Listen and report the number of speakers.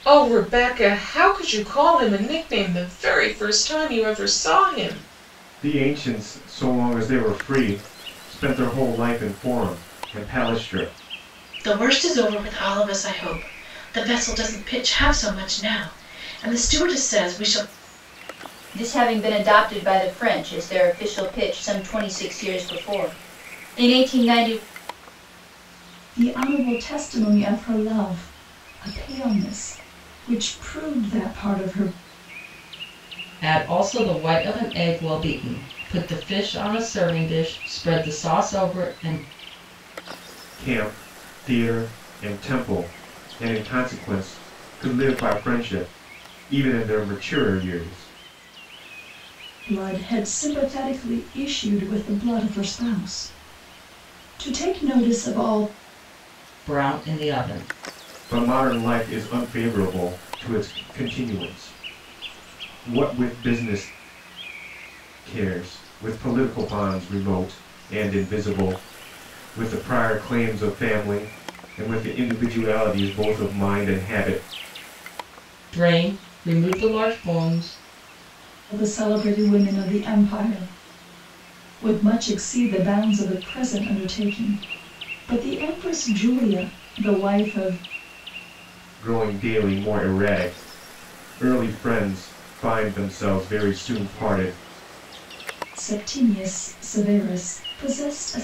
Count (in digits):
6